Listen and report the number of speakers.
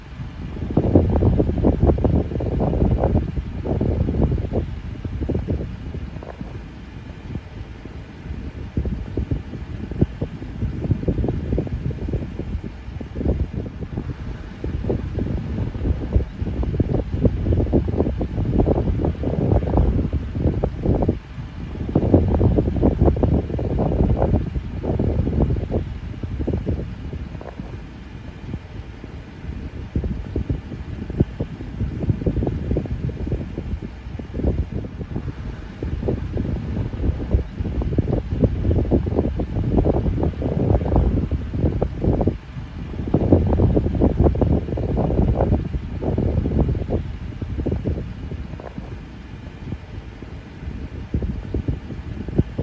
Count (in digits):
0